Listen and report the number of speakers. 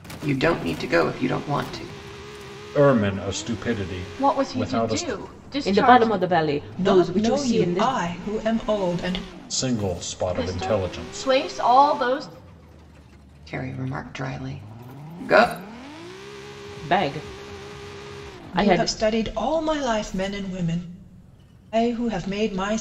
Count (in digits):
5